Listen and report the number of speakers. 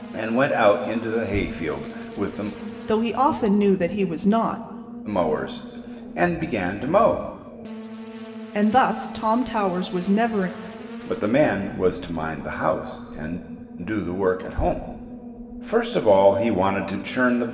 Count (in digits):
2